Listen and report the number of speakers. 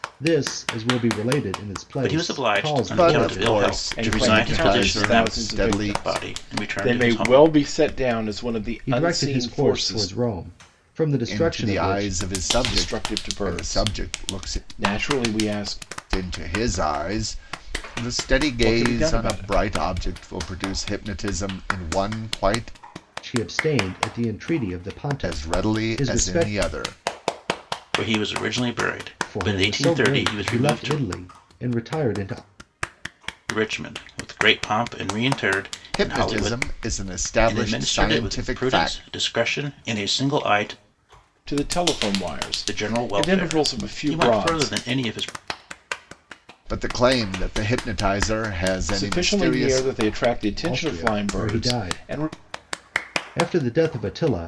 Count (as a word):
four